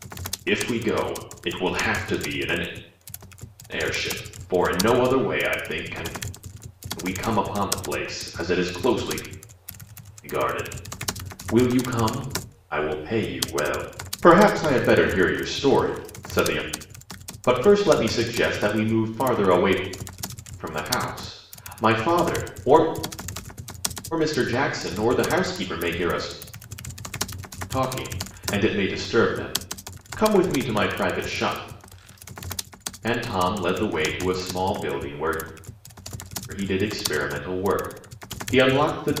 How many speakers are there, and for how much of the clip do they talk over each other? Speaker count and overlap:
one, no overlap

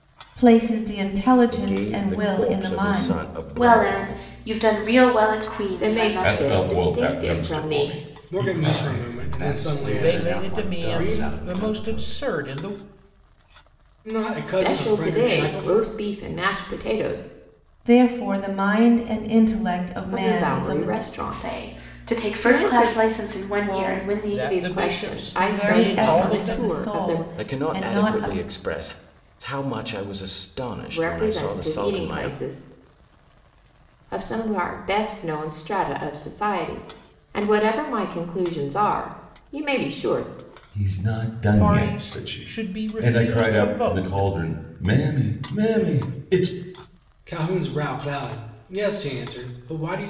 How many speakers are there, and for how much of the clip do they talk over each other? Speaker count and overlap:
eight, about 43%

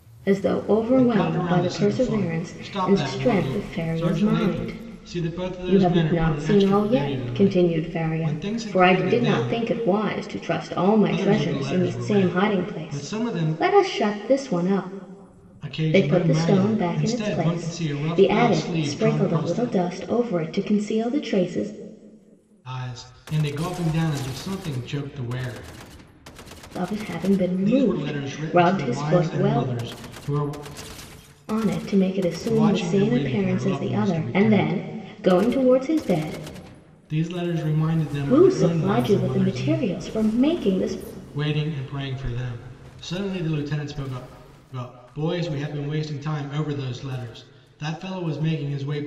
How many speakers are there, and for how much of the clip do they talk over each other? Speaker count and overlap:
two, about 42%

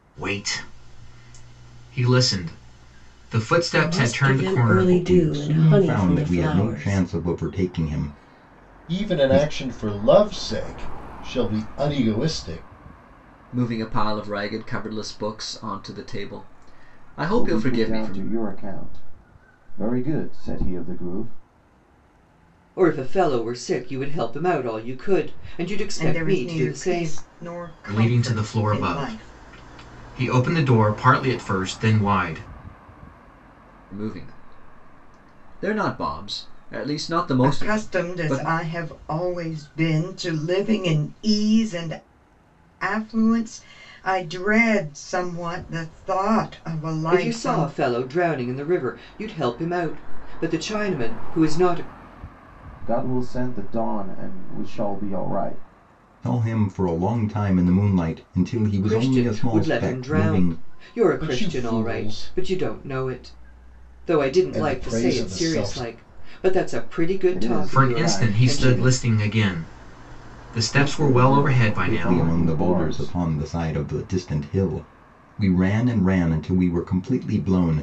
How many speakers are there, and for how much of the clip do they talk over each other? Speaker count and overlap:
eight, about 25%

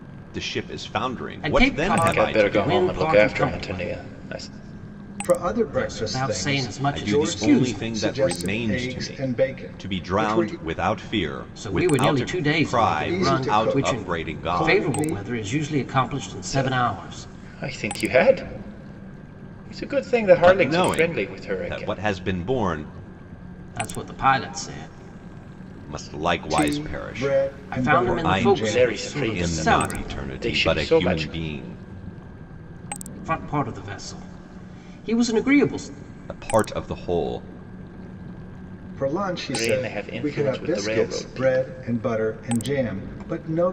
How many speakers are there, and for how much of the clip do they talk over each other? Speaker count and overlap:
four, about 46%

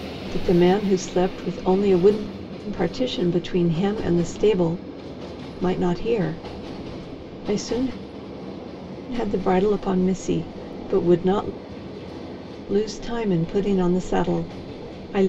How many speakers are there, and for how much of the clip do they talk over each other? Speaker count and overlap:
one, no overlap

